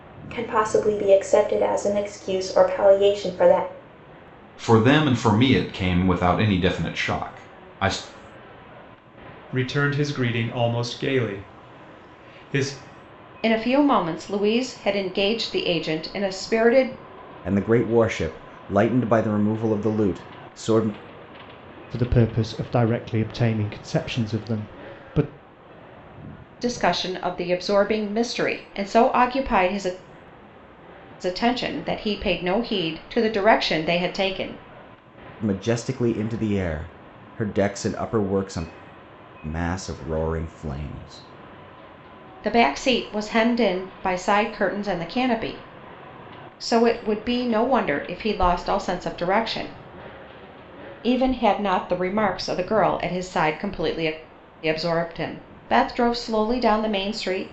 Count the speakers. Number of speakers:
six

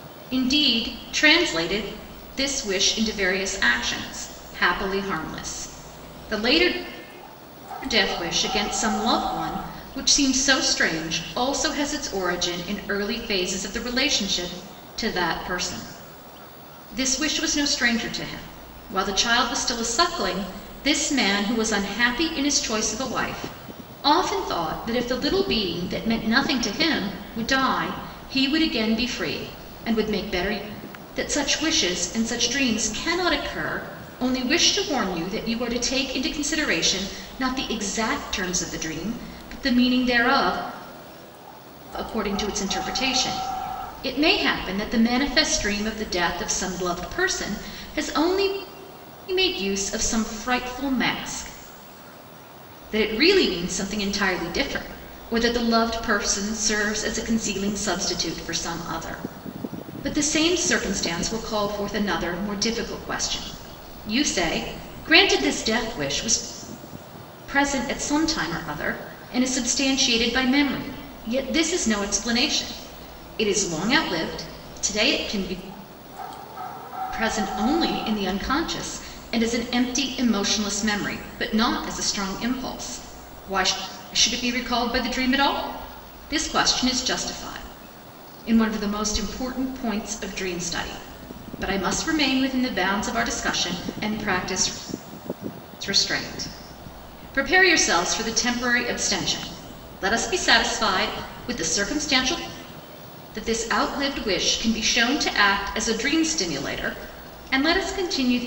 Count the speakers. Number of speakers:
one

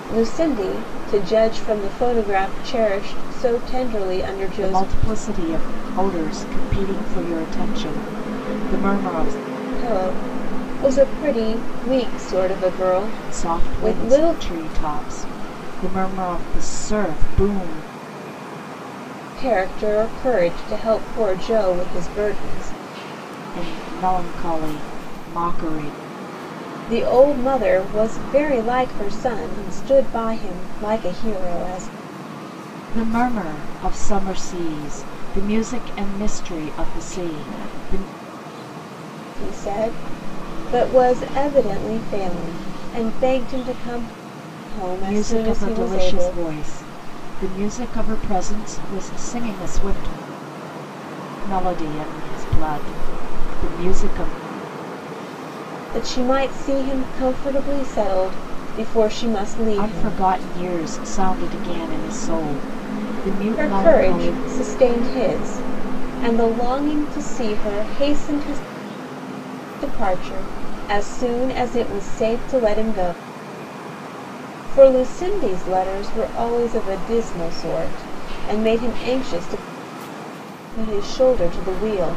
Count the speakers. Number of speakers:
two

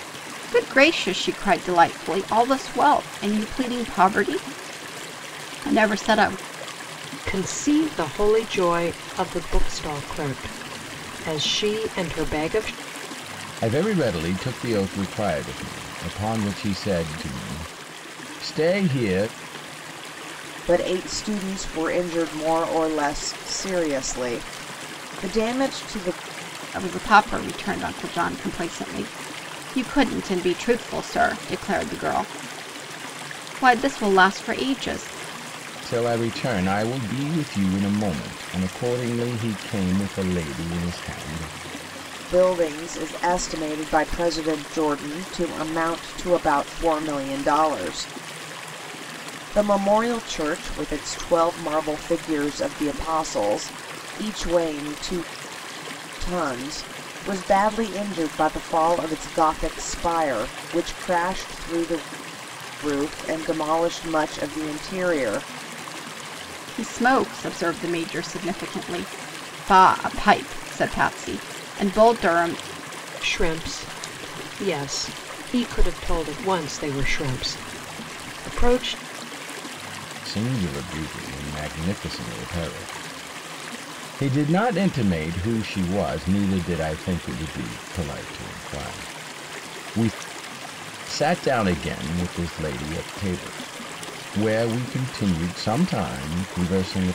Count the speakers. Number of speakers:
four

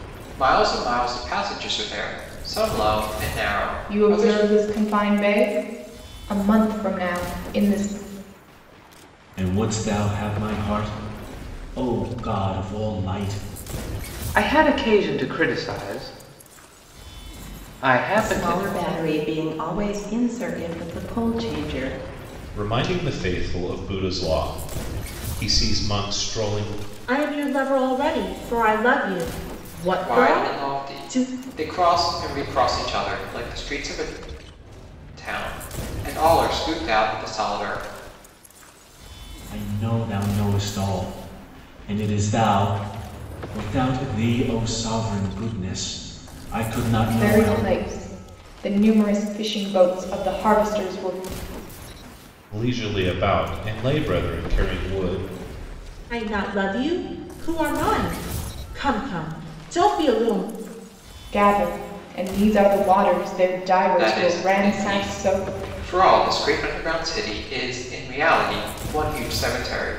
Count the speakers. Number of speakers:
seven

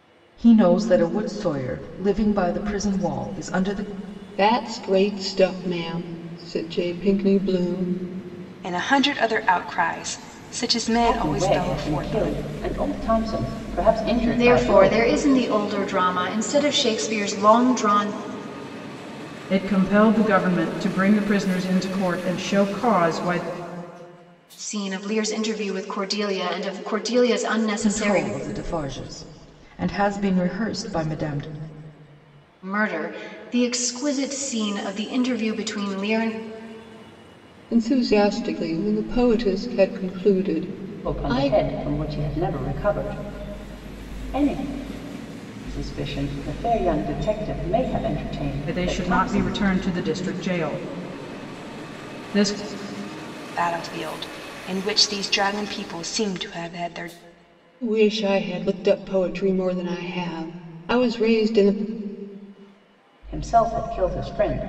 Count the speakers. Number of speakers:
six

